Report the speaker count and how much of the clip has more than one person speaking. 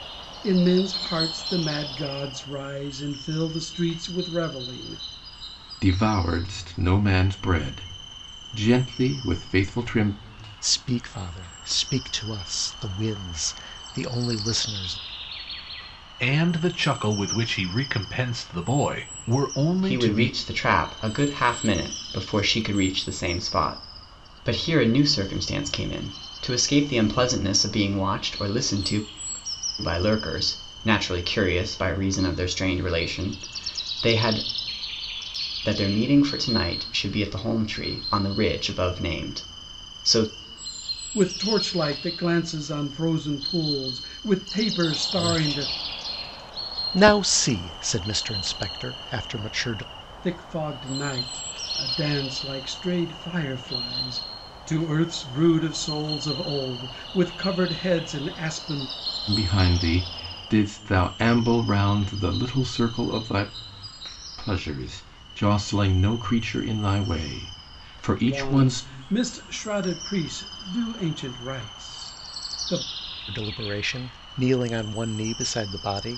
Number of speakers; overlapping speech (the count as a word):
five, about 2%